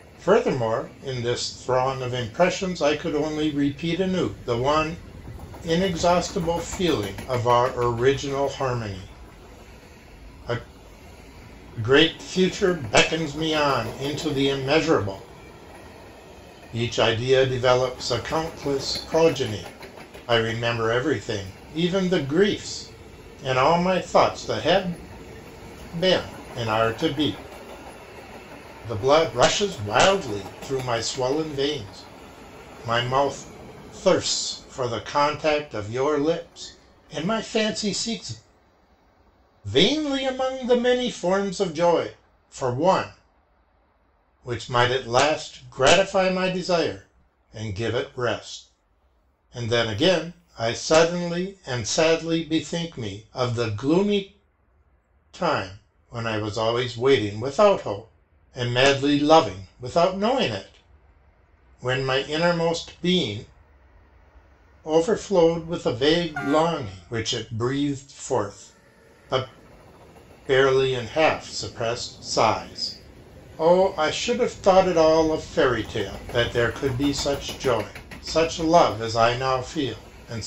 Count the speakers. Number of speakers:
one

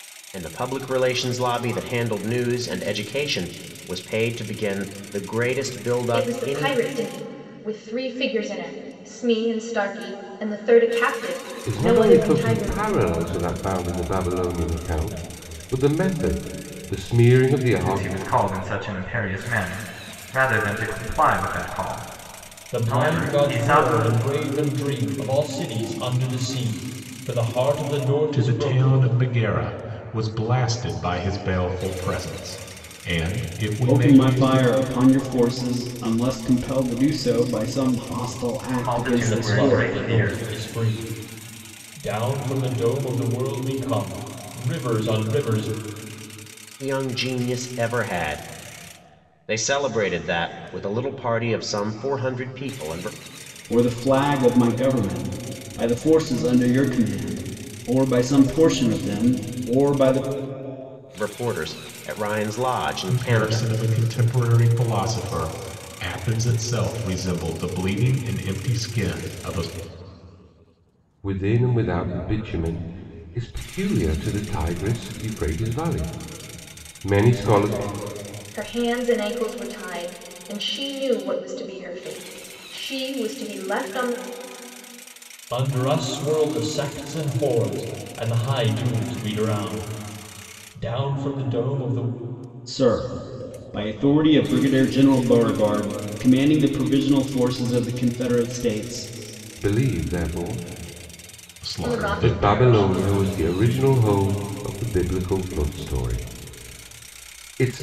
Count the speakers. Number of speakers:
seven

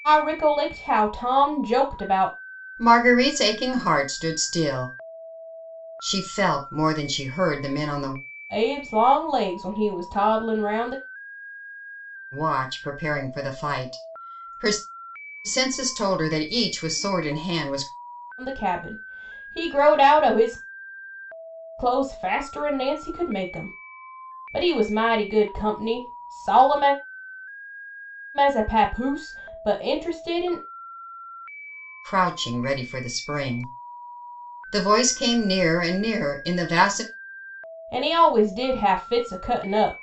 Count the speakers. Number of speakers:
two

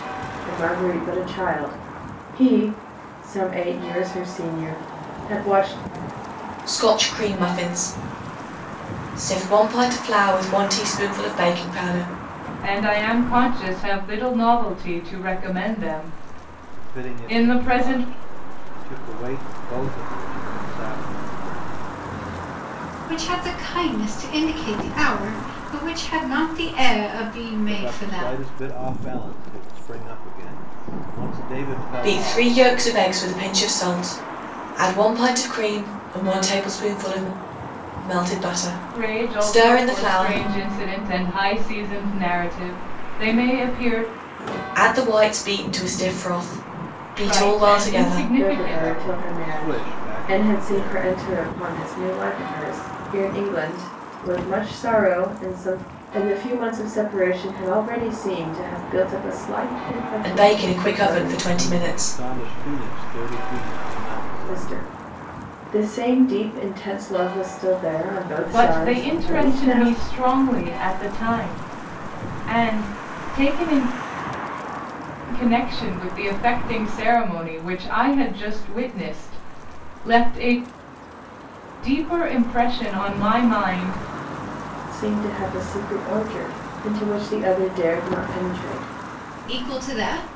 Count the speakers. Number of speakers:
five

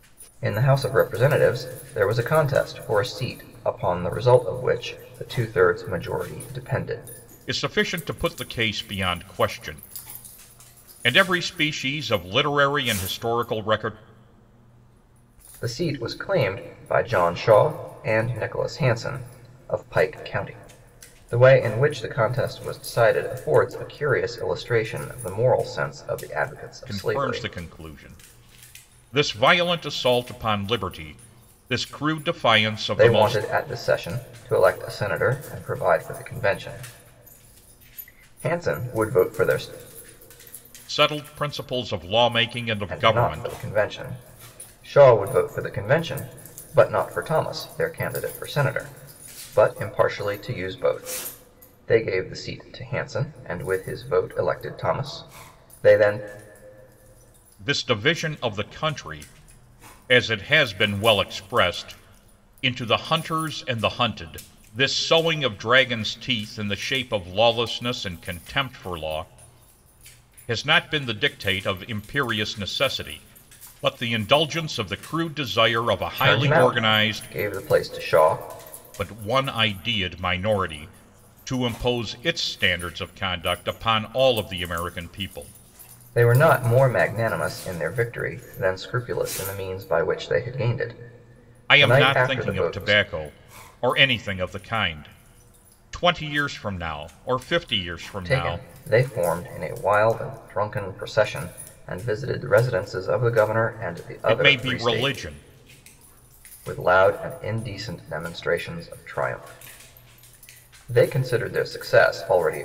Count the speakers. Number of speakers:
two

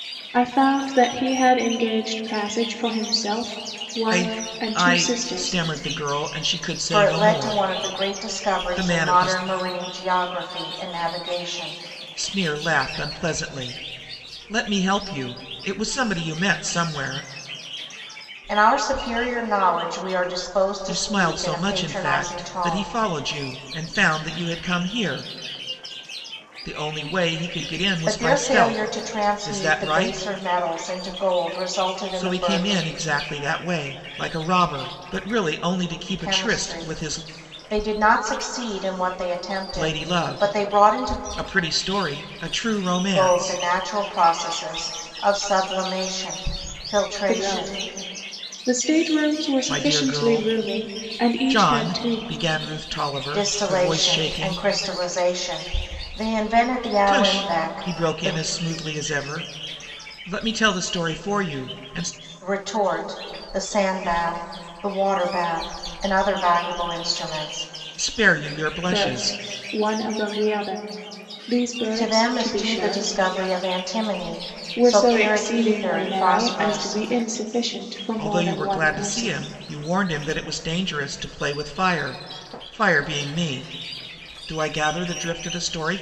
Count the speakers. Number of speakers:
three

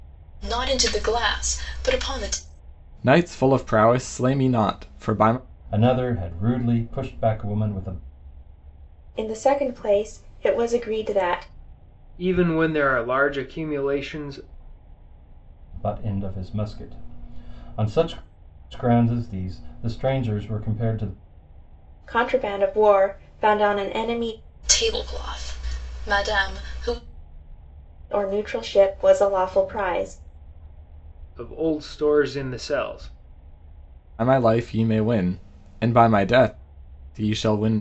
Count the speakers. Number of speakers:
five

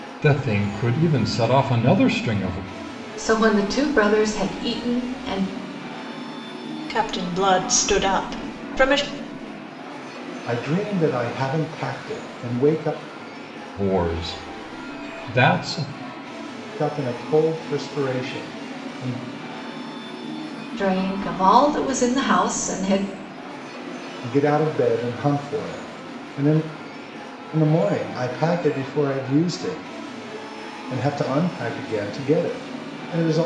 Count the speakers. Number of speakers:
four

